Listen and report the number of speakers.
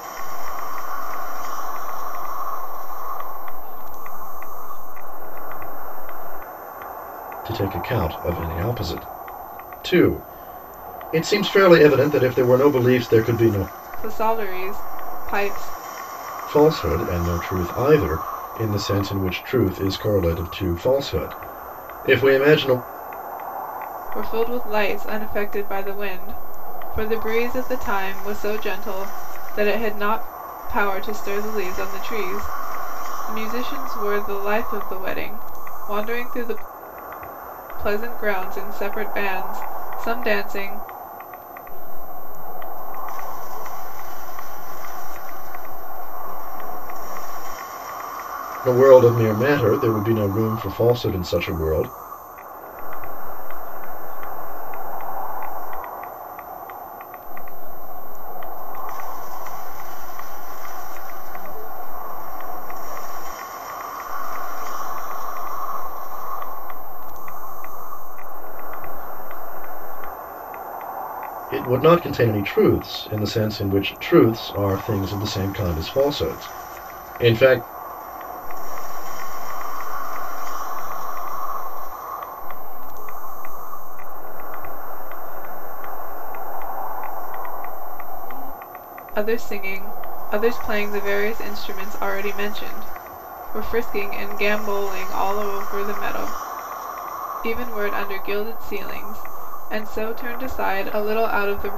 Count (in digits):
3